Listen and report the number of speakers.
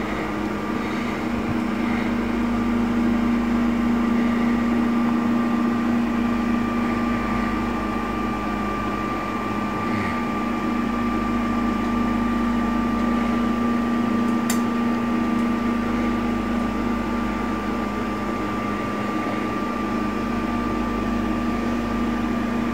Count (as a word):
zero